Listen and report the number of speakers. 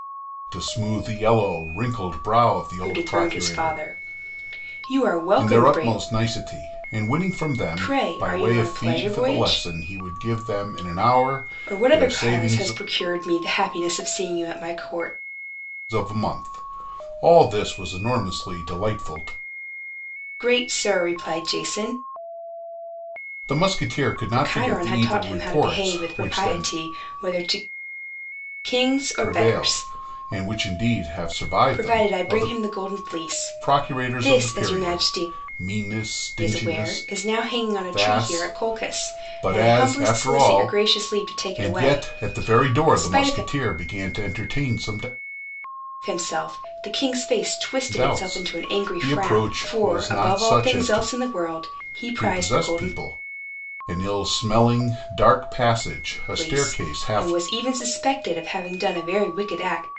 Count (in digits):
2